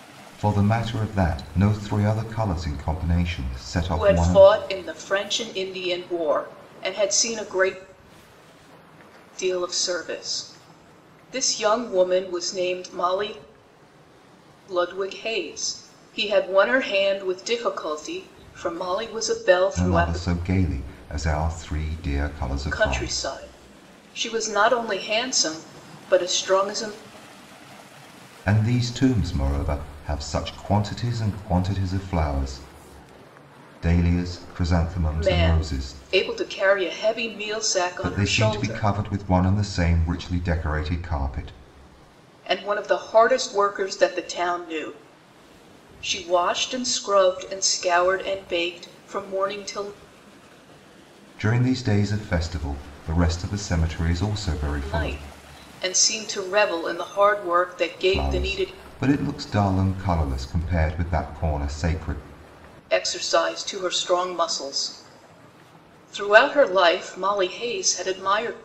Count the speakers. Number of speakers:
2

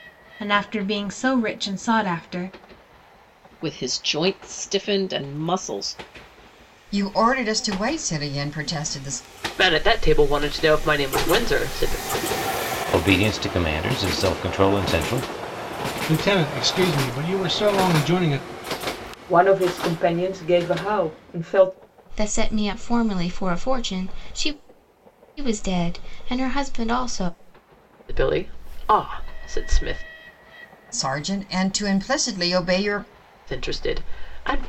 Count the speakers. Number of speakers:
8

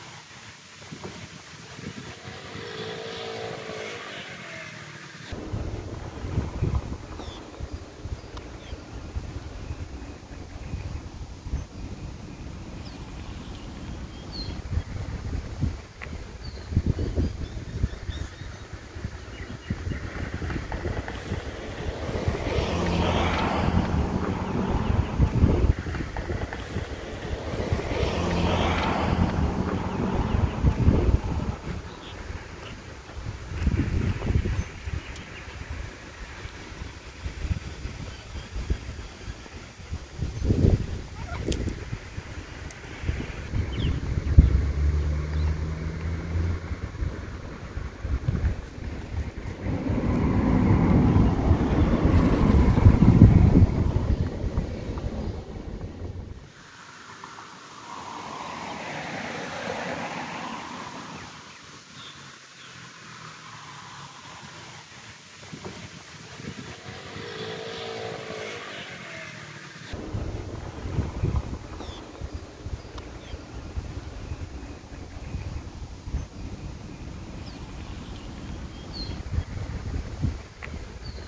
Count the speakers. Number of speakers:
0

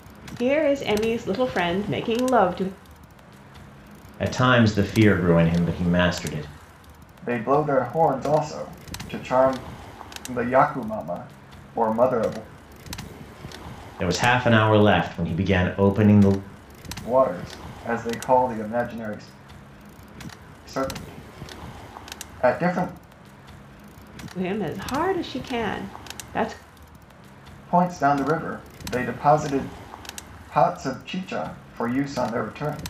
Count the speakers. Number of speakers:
3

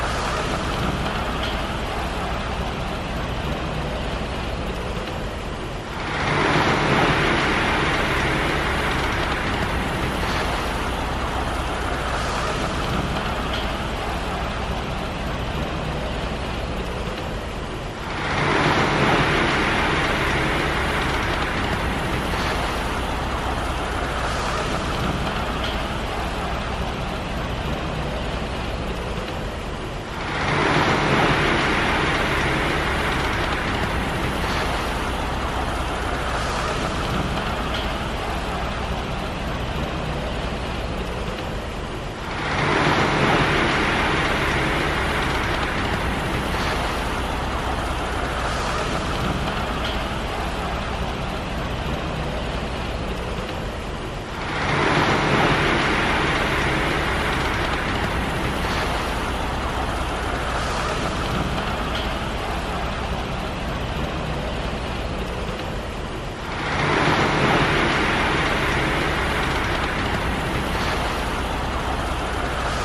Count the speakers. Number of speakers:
0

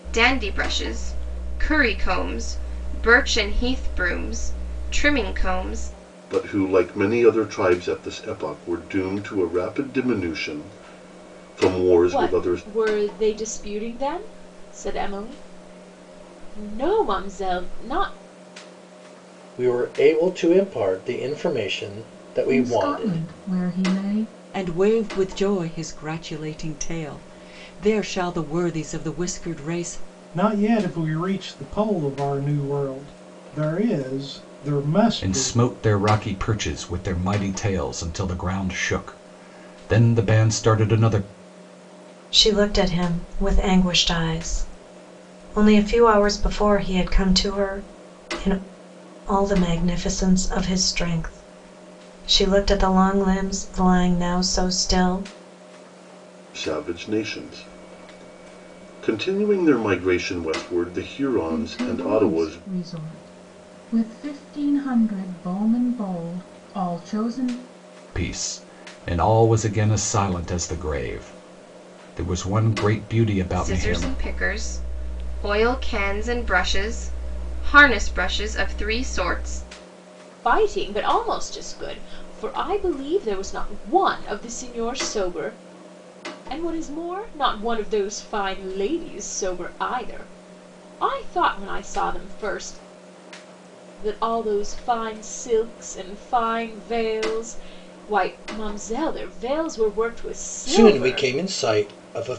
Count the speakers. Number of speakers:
9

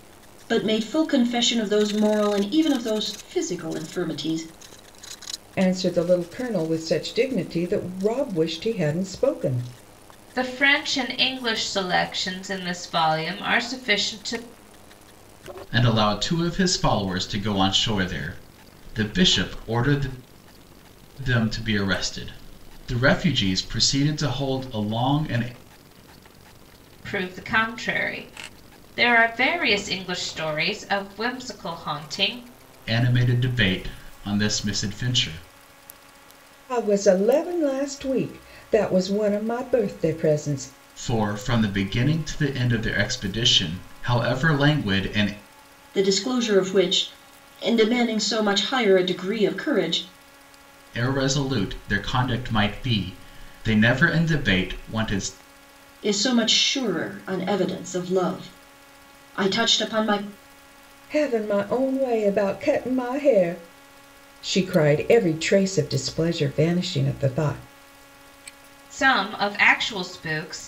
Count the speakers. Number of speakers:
4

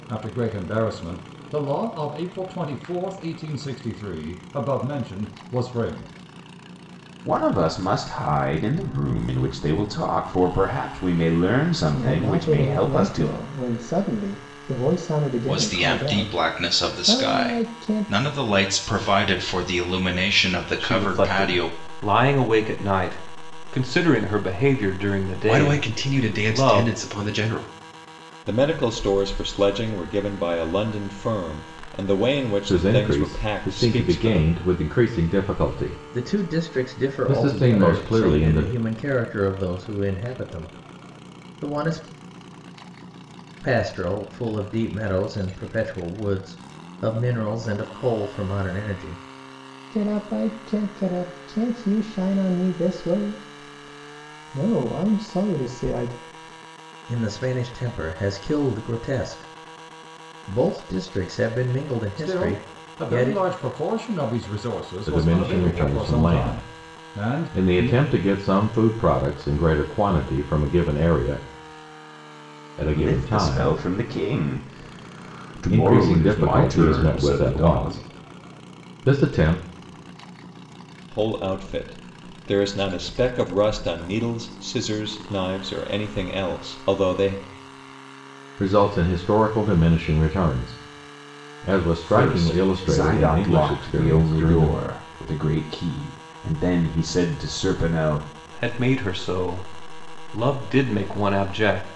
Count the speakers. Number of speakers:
9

